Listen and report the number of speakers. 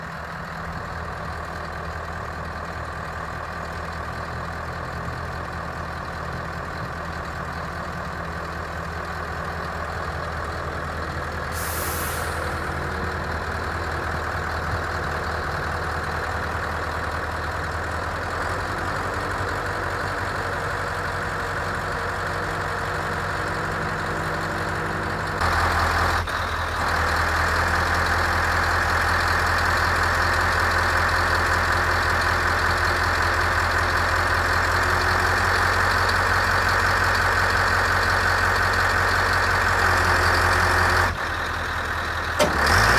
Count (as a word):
zero